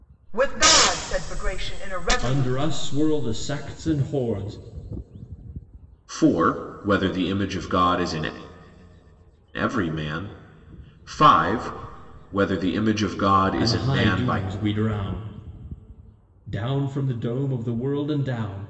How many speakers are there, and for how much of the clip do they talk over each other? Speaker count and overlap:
three, about 8%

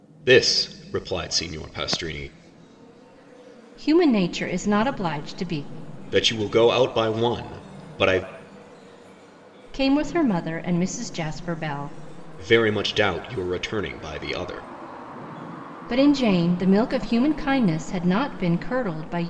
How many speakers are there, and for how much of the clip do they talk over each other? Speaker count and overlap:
two, no overlap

